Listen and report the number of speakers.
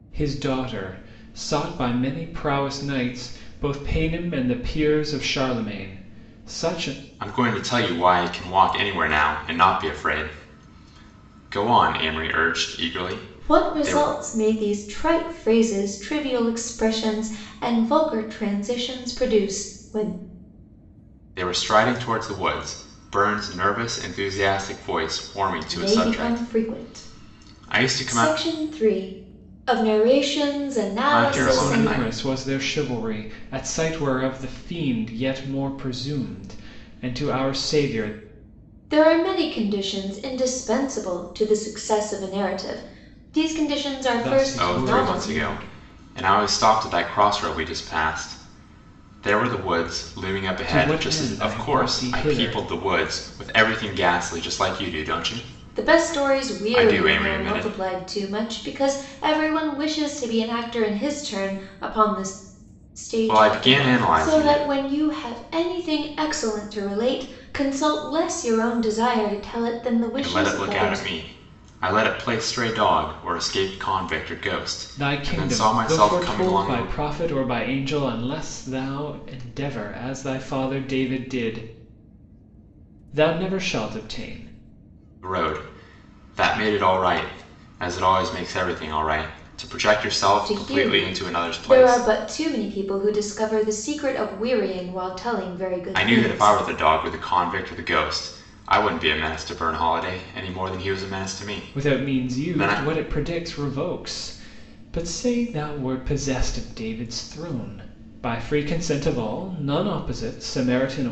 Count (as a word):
three